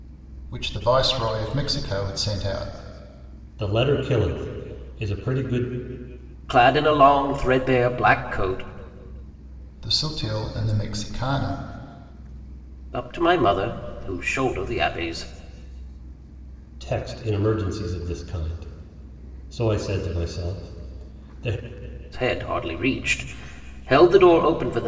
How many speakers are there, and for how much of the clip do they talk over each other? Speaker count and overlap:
3, no overlap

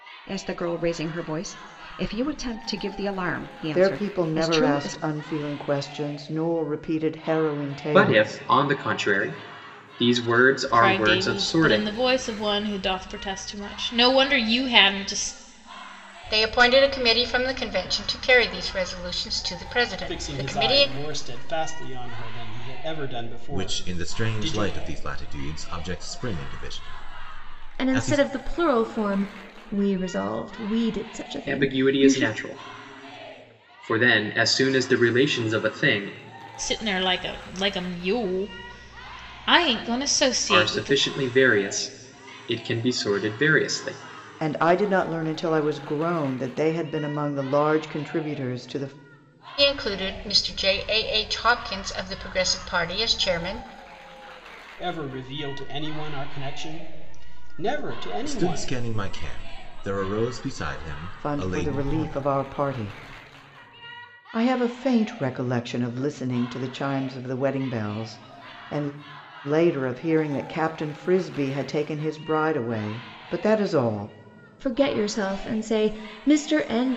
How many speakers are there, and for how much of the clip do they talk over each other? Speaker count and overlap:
8, about 12%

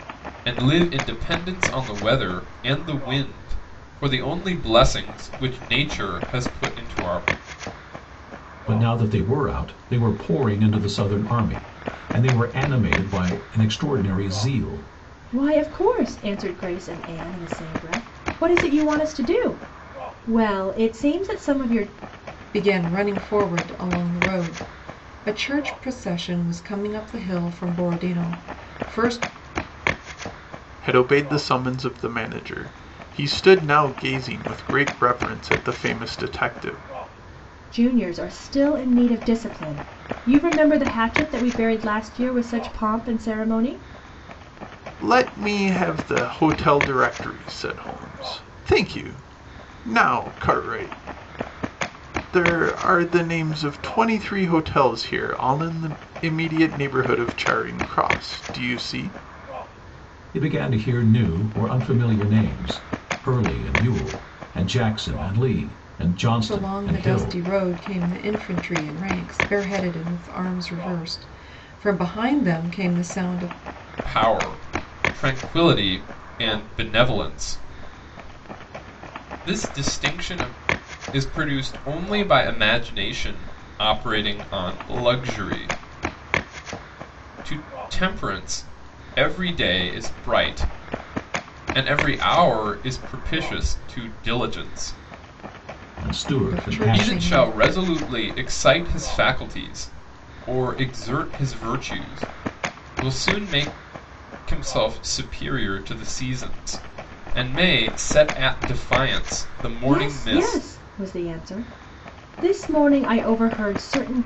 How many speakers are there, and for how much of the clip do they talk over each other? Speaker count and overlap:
5, about 3%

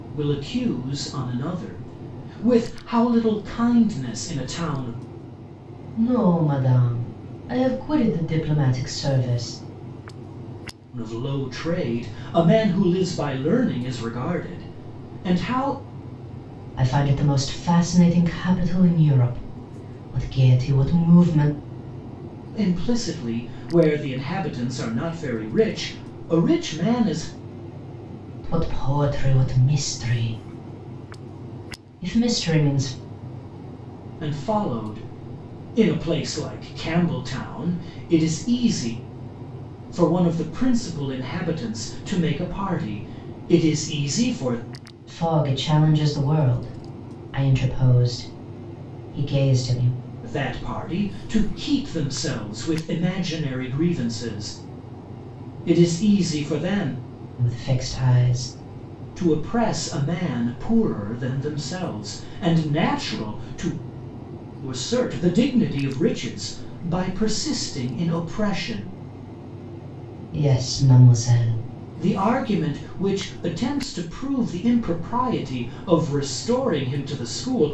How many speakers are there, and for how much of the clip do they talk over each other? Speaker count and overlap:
2, no overlap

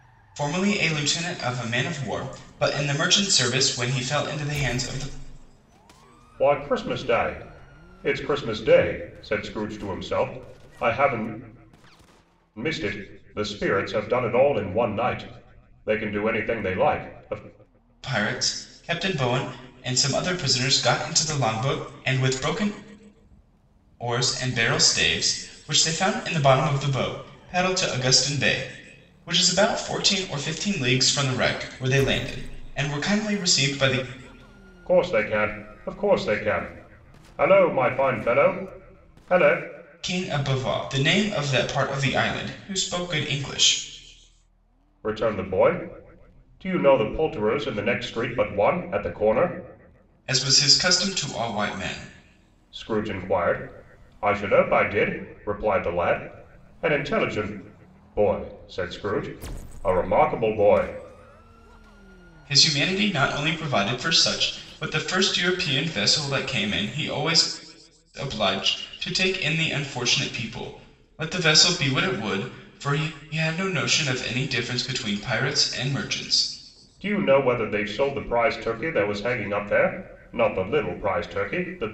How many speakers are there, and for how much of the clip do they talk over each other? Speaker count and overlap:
2, no overlap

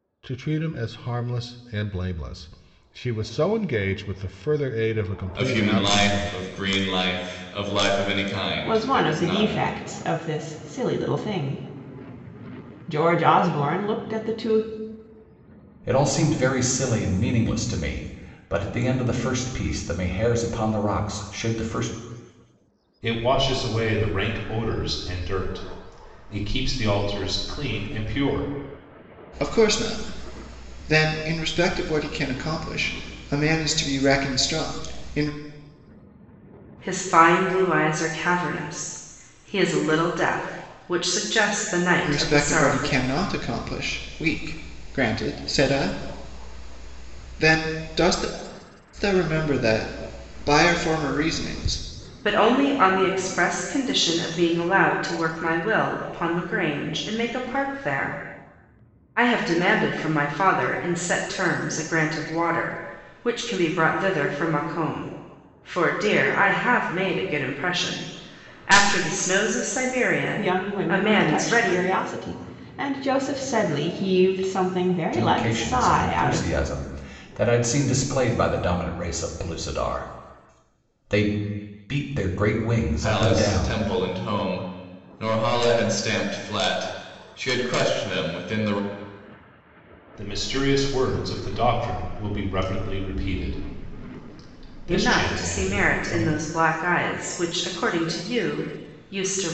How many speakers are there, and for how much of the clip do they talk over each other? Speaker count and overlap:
7, about 8%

